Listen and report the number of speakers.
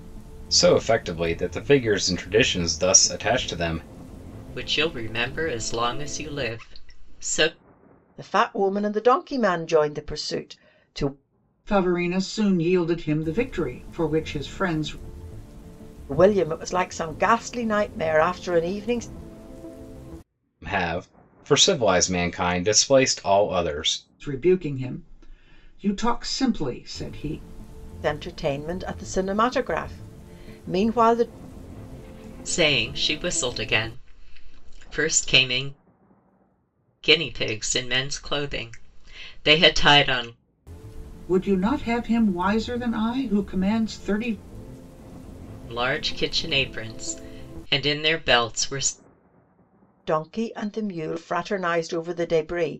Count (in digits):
4